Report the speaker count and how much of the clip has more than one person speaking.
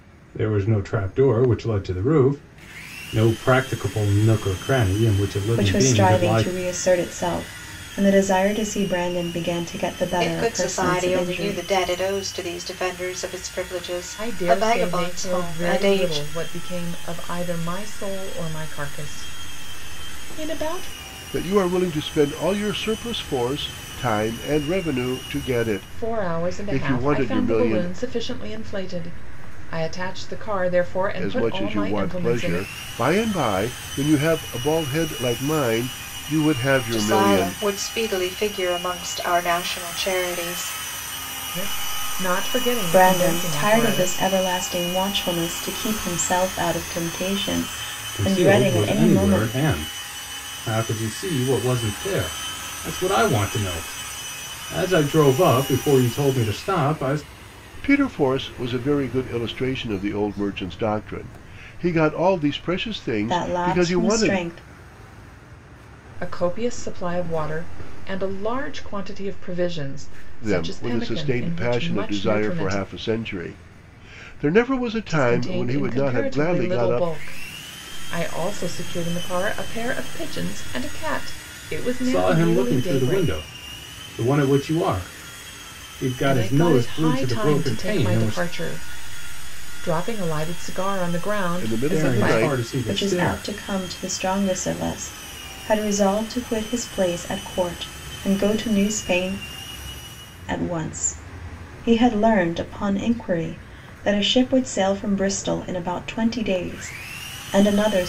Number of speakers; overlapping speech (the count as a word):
five, about 21%